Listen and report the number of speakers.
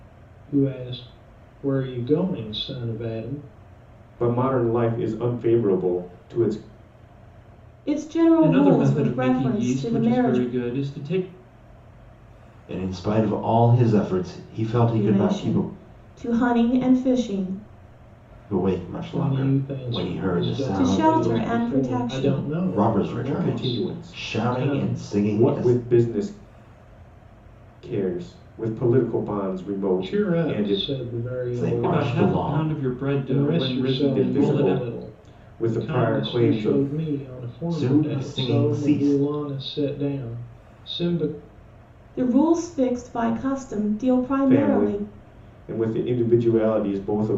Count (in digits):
5